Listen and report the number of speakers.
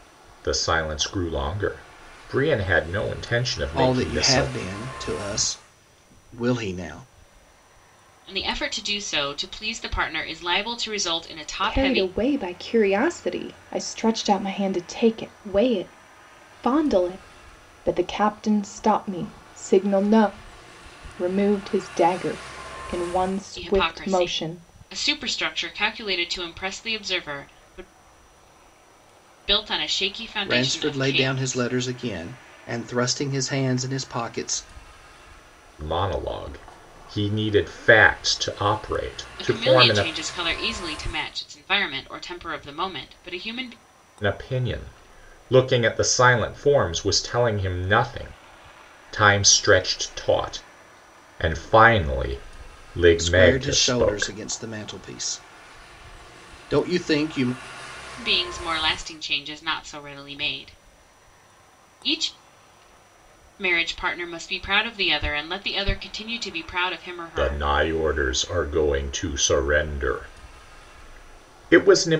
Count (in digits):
4